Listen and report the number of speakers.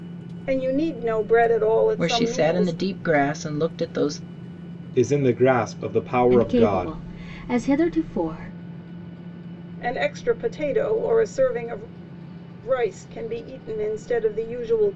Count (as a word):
four